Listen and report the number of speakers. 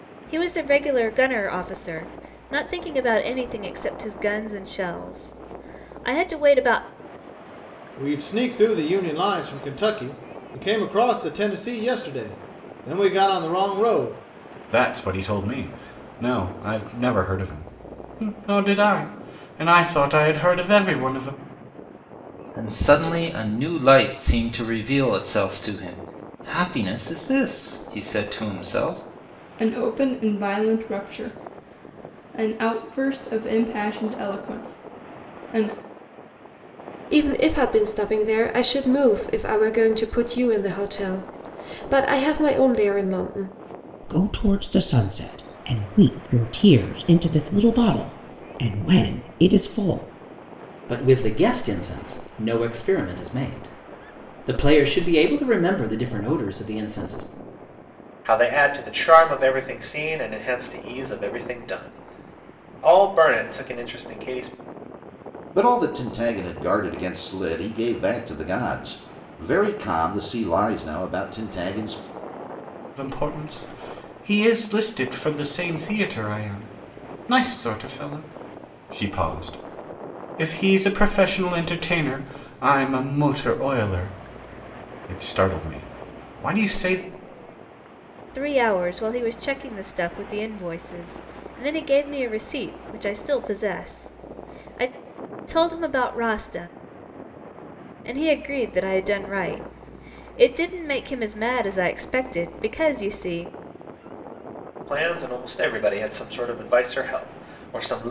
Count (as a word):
ten